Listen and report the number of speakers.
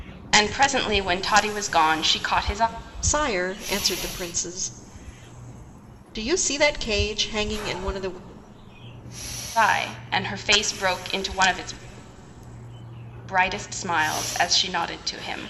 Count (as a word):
two